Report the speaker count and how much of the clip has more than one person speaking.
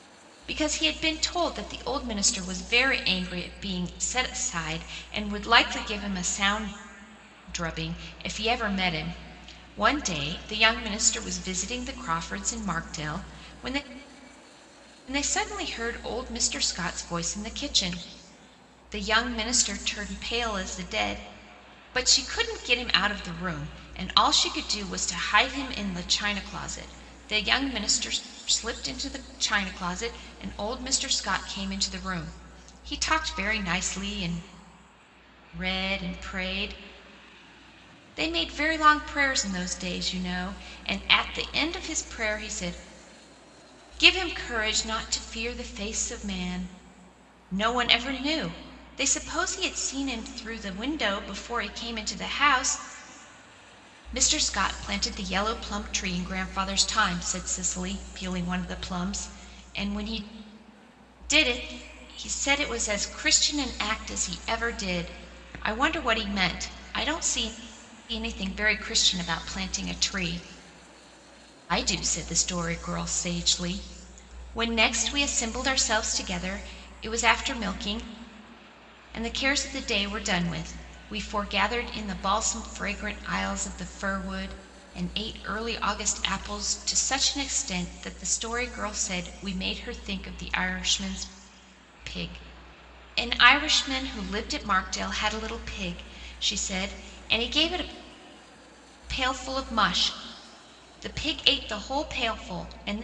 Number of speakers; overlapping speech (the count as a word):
one, no overlap